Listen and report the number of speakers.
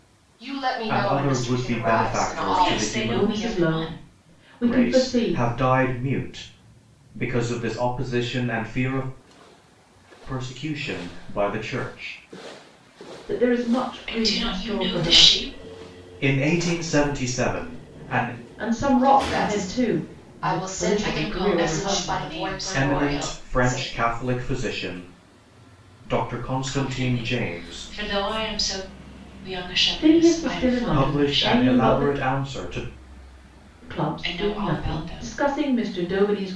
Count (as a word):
four